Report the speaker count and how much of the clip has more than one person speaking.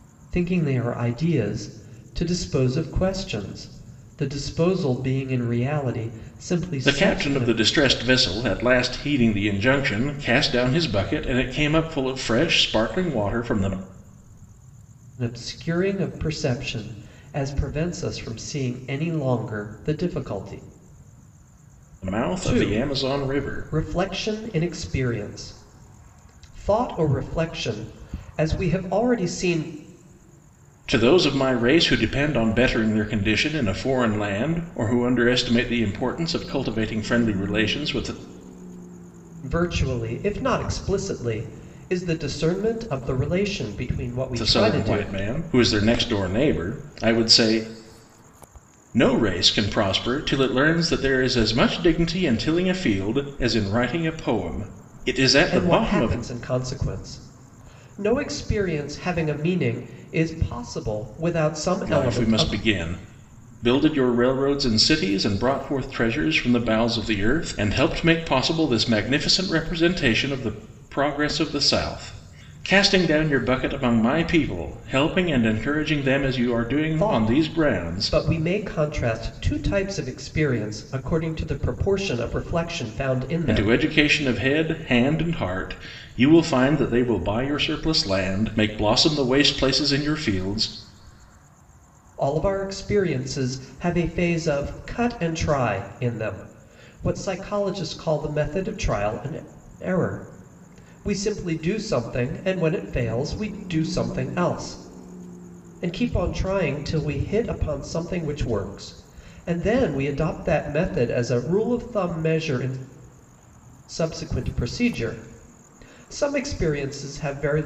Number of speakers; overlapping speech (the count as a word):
two, about 5%